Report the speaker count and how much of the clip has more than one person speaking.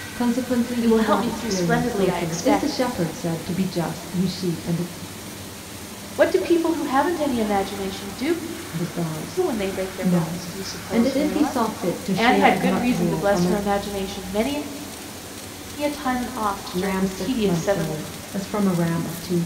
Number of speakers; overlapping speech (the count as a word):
two, about 35%